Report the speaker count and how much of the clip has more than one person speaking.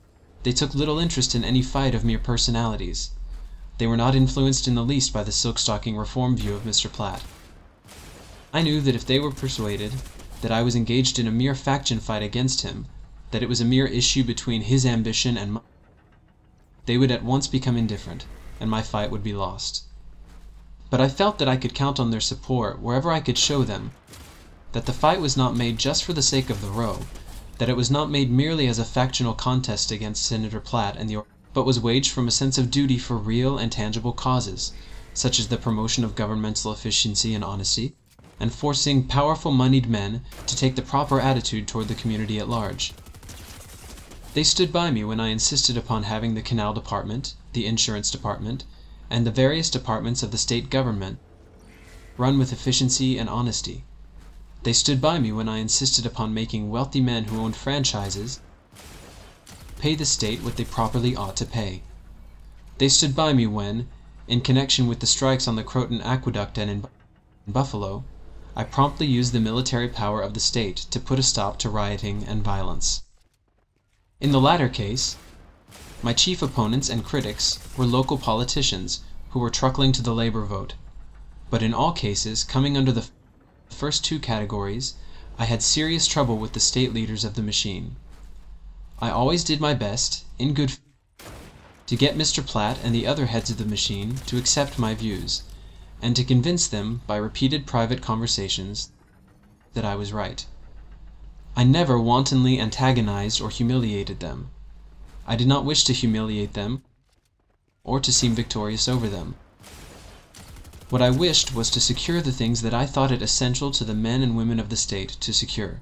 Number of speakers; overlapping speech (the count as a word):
one, no overlap